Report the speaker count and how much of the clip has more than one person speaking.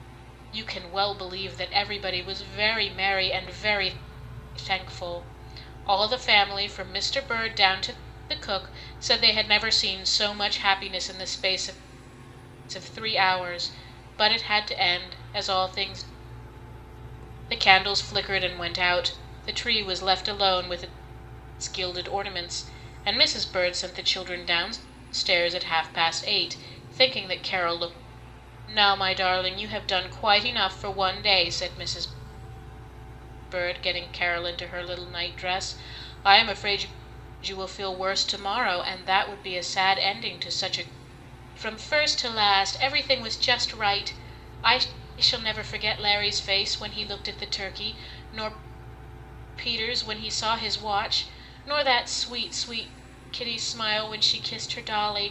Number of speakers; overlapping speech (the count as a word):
one, no overlap